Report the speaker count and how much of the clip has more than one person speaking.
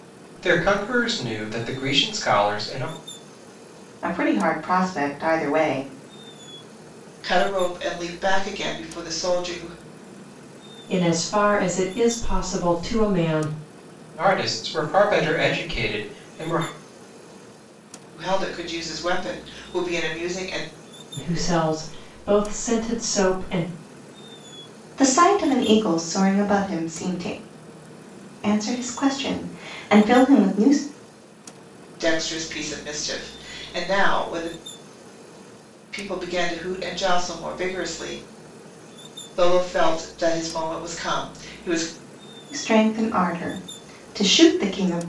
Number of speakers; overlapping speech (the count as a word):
four, no overlap